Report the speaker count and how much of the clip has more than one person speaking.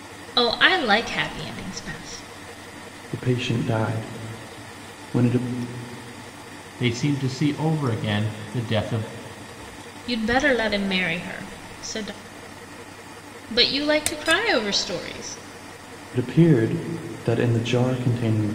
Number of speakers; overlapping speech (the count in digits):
3, no overlap